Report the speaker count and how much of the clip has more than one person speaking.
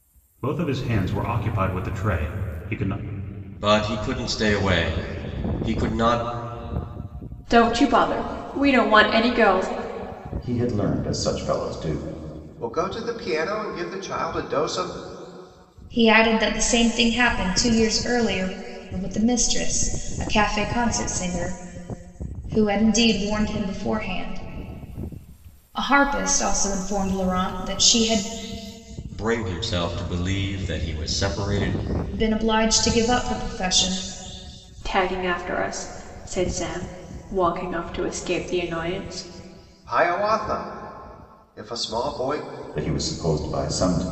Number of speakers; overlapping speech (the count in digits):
6, no overlap